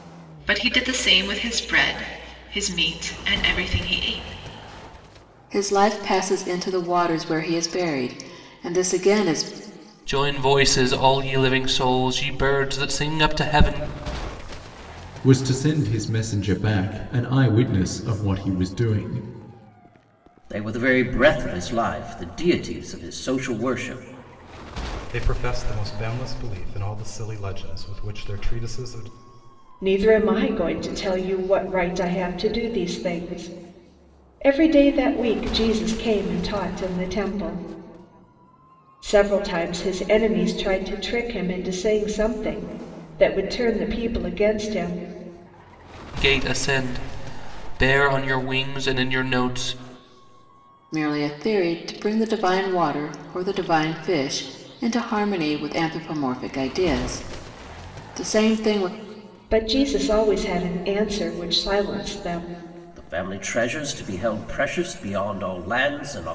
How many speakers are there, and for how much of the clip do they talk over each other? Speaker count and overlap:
seven, no overlap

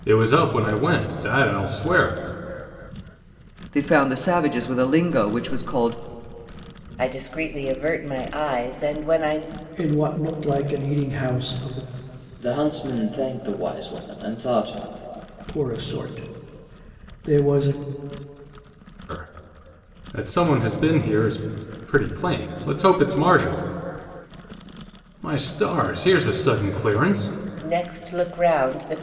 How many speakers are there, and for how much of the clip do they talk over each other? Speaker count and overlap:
five, no overlap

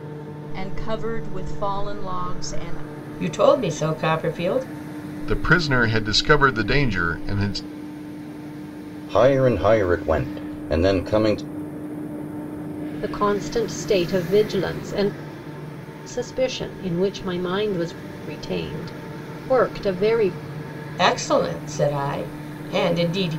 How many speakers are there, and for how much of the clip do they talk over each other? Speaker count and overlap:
five, no overlap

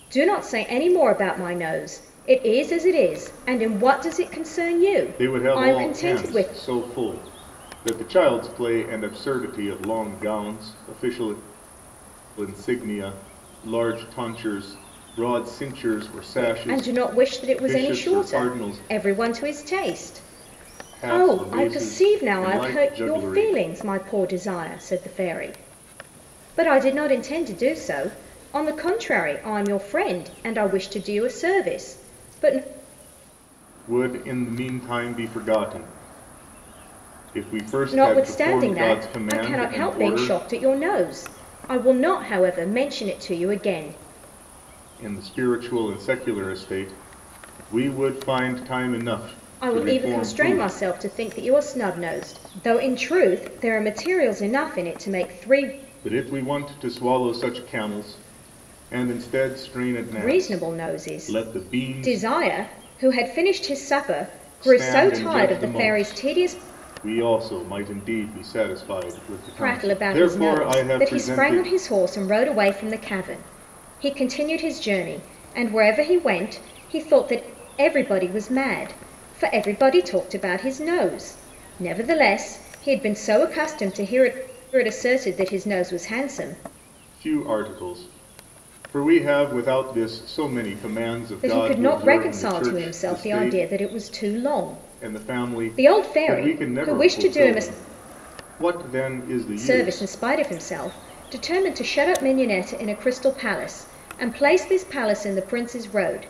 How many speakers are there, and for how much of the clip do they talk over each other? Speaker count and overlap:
two, about 21%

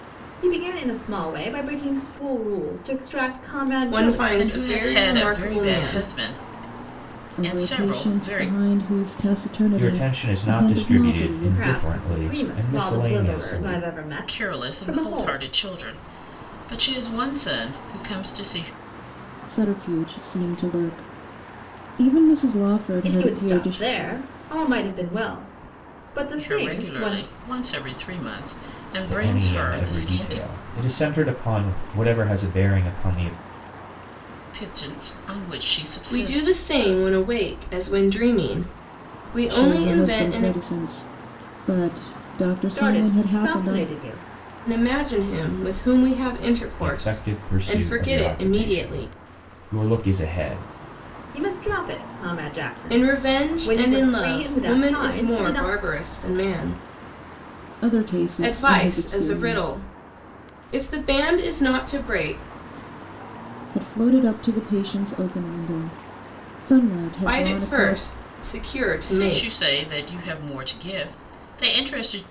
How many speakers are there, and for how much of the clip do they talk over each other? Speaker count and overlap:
five, about 31%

